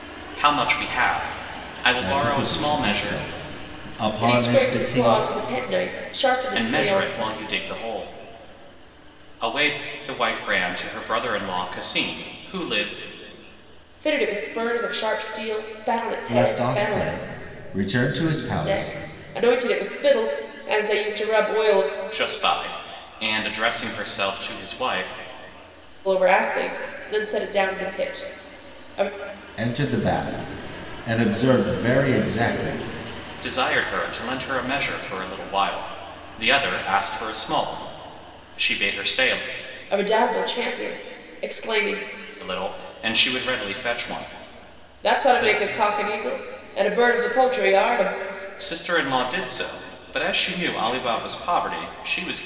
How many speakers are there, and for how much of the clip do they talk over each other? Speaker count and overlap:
3, about 9%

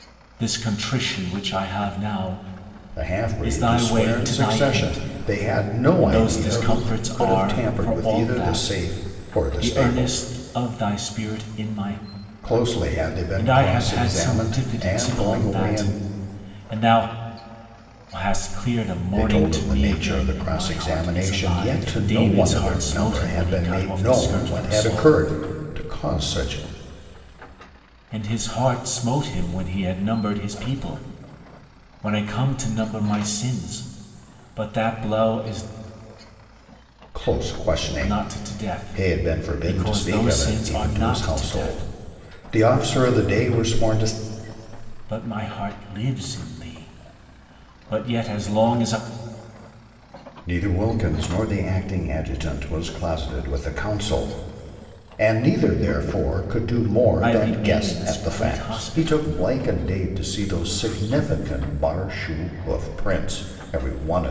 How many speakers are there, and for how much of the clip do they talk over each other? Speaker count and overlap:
2, about 34%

